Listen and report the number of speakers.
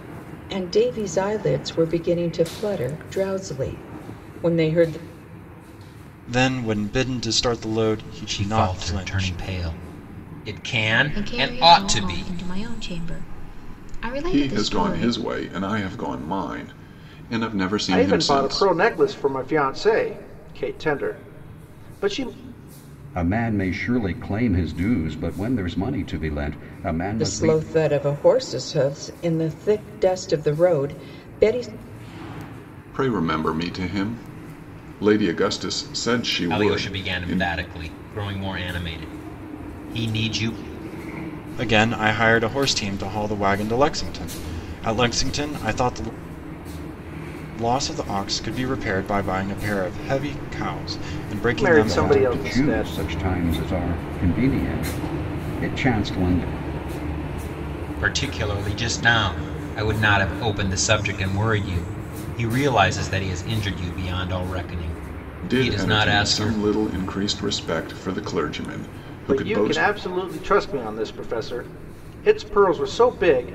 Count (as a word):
seven